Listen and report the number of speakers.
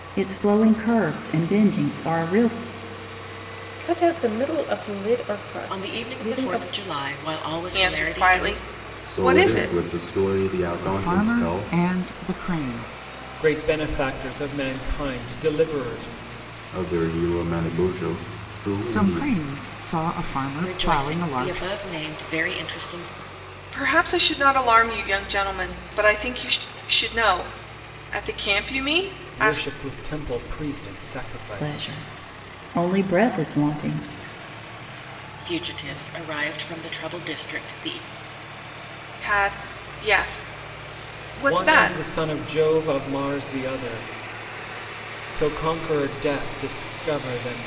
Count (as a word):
seven